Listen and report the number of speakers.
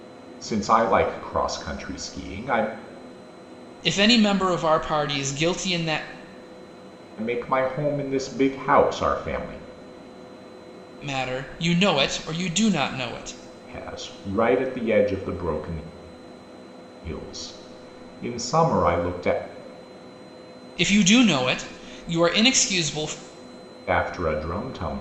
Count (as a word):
two